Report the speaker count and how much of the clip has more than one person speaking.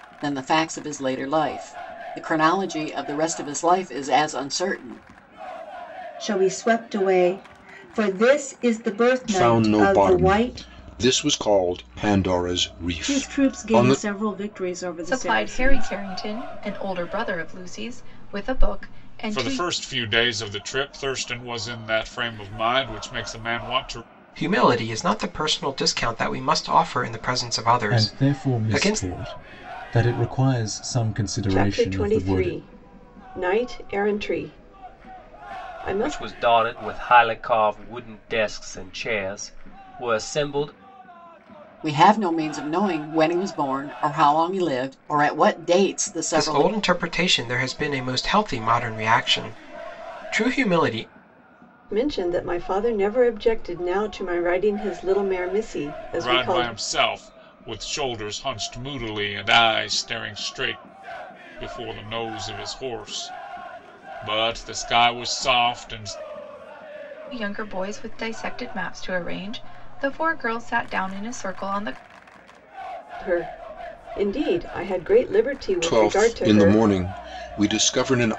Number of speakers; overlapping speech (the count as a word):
ten, about 11%